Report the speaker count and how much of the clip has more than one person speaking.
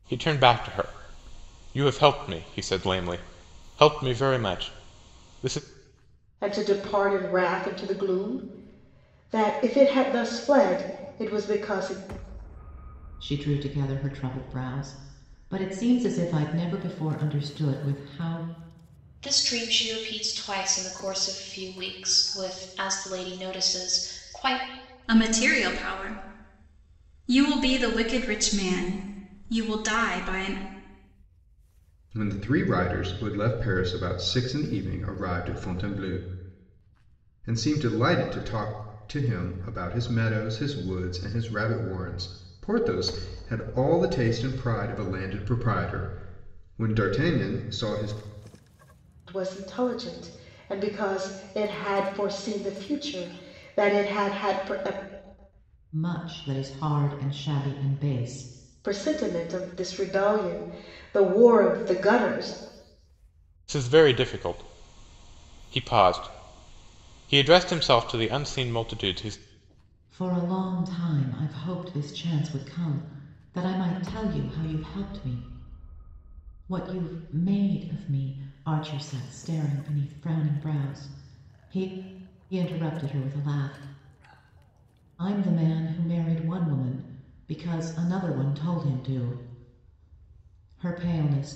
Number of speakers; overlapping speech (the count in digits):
6, no overlap